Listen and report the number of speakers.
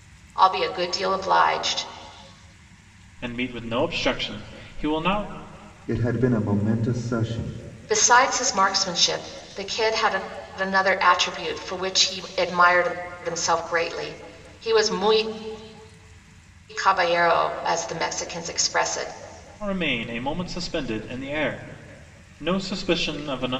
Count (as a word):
three